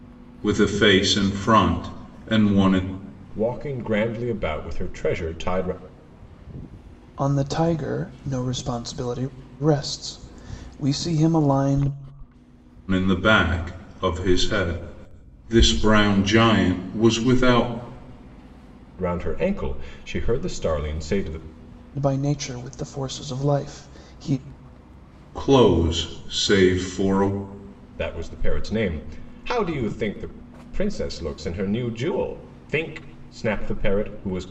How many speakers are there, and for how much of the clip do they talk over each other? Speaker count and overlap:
3, no overlap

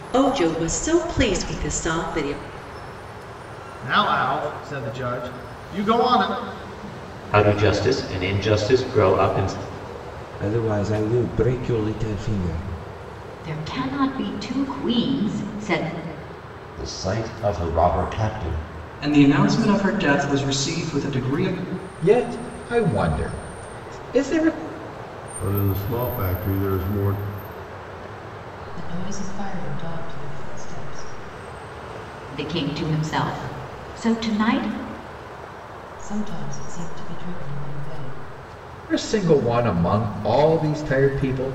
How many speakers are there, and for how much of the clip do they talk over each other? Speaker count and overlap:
10, no overlap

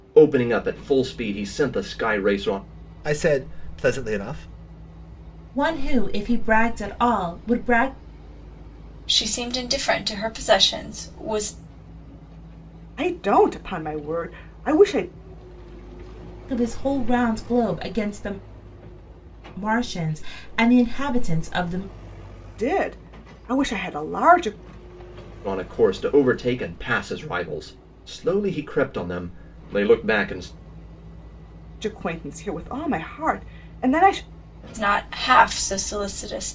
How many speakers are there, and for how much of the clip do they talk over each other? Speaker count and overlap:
5, no overlap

